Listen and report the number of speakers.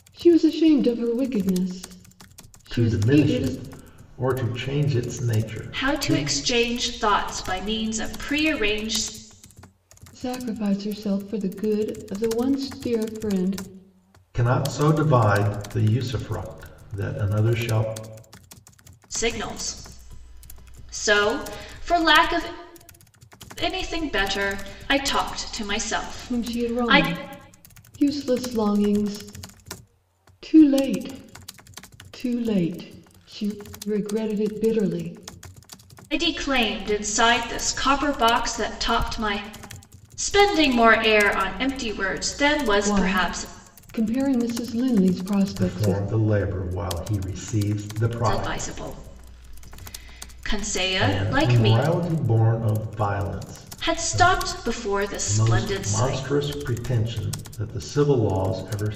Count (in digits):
3